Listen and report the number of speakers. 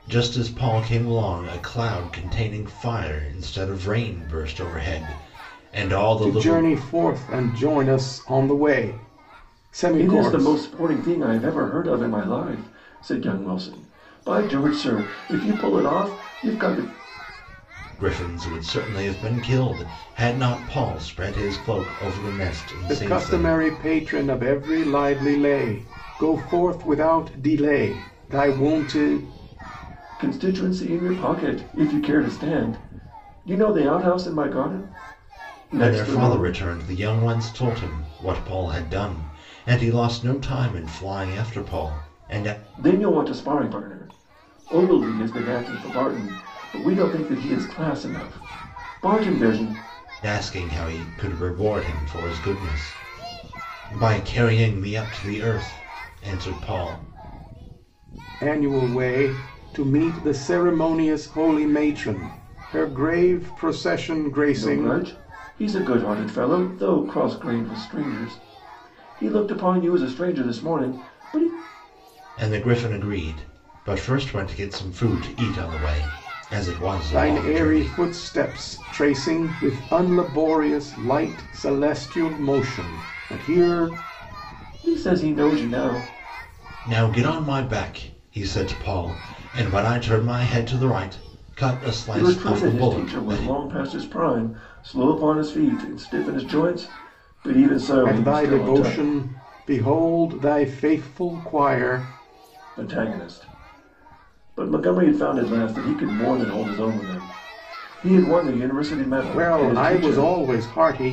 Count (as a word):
three